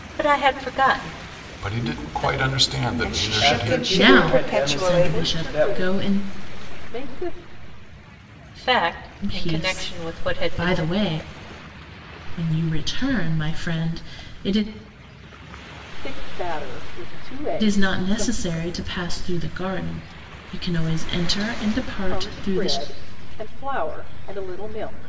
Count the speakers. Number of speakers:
6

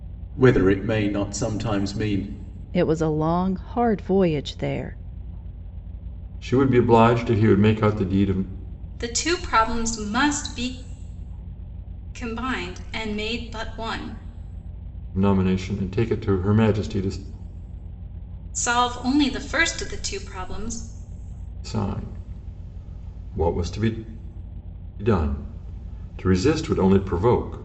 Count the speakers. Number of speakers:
4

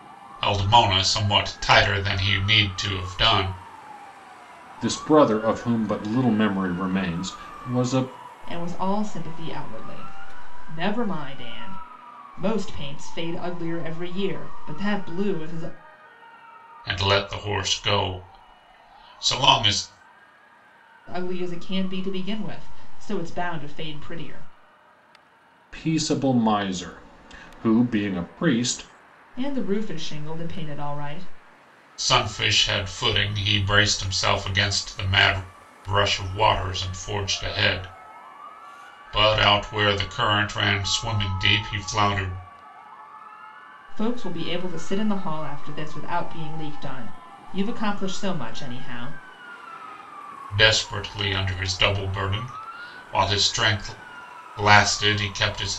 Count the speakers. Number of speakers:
3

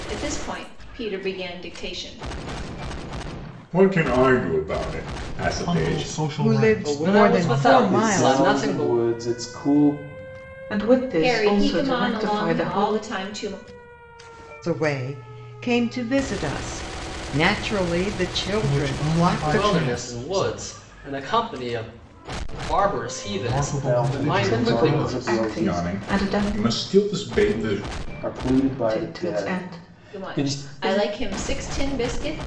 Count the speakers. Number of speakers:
7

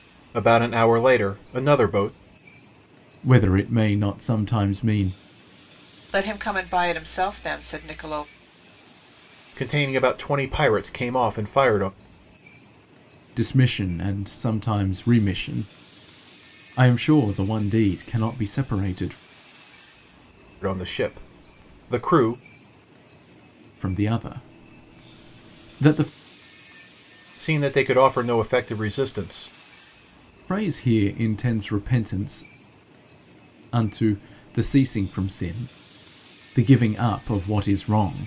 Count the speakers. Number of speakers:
3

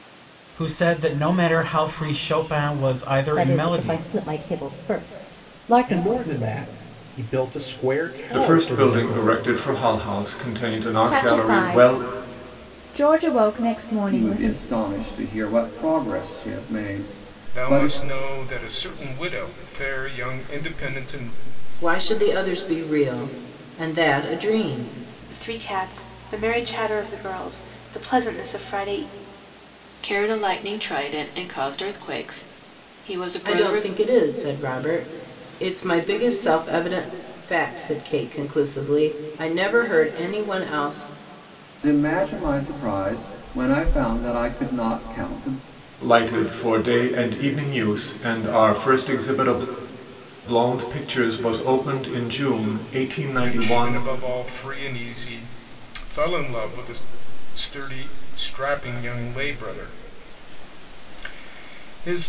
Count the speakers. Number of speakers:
10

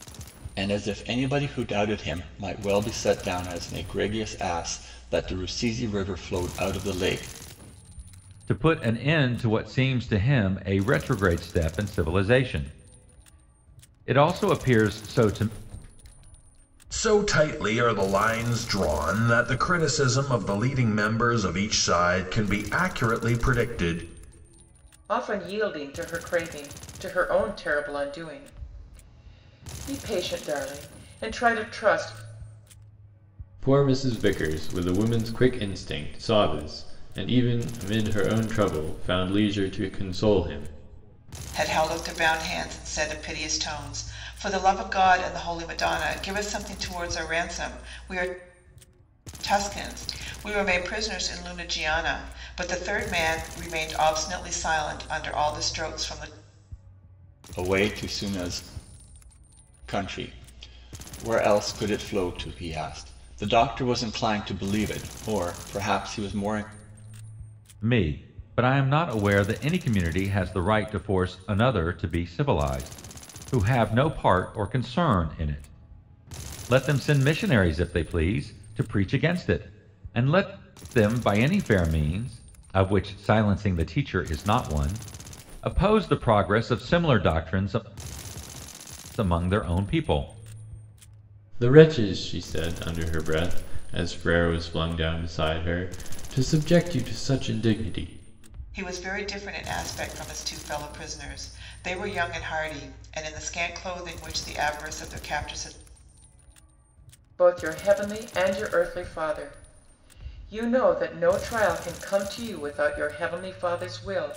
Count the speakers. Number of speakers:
6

